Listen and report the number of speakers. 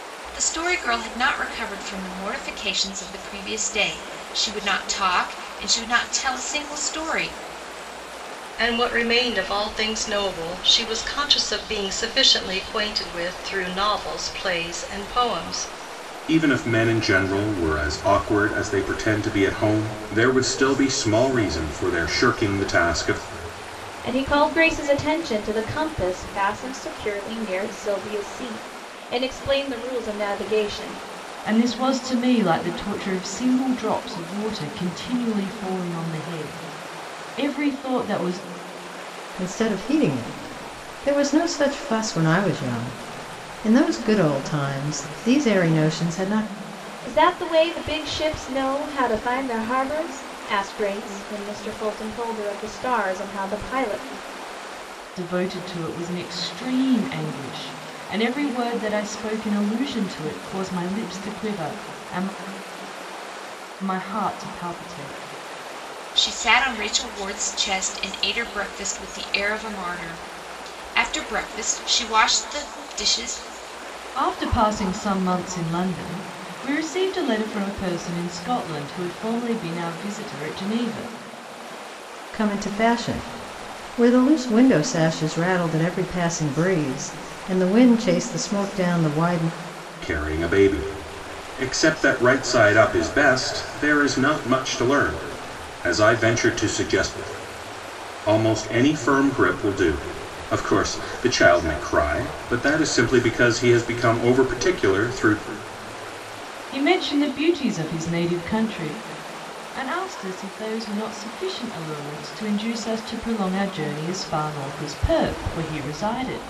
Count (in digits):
6